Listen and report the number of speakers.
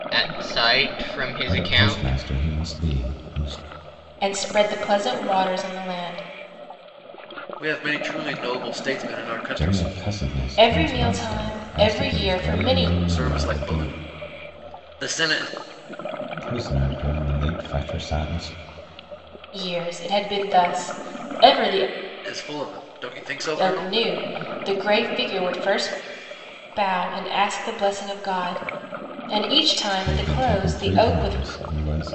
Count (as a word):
four